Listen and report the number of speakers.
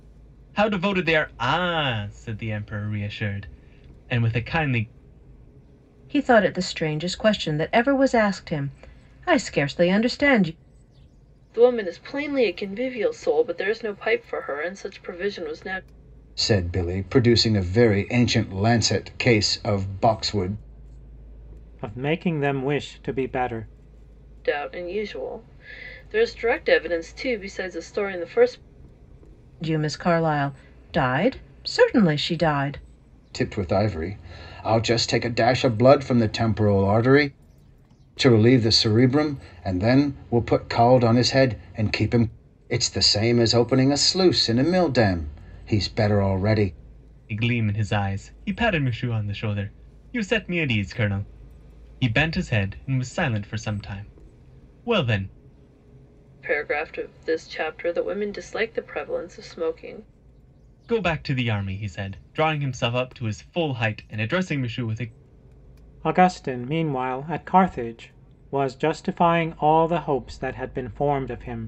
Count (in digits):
5